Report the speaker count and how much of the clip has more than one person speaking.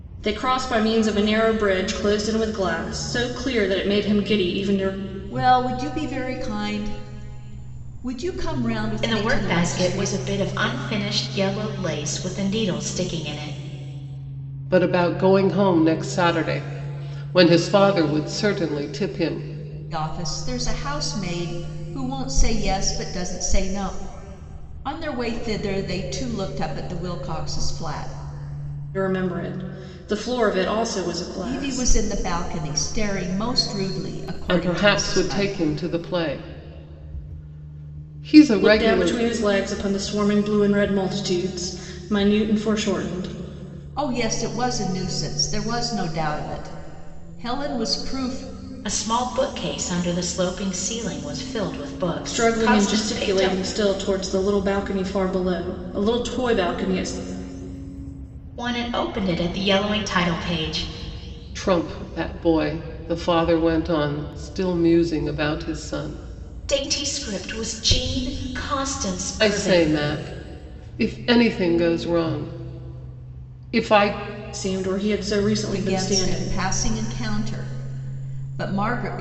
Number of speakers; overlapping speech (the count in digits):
4, about 8%